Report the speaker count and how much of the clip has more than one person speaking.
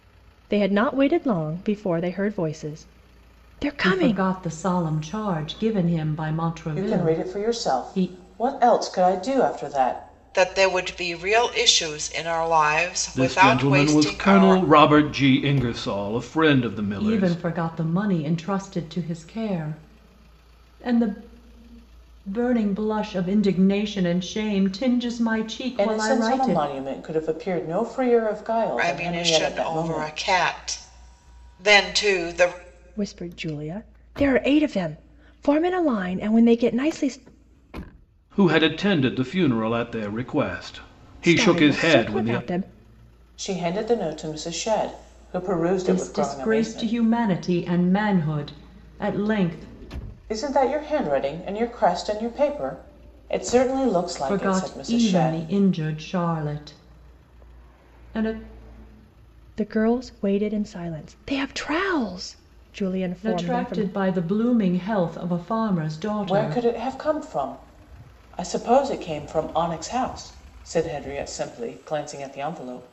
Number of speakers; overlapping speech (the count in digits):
5, about 15%